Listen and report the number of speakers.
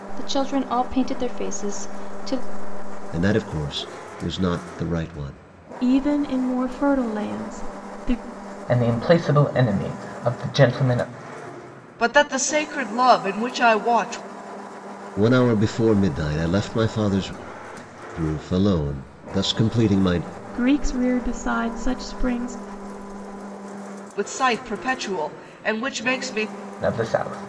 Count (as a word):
five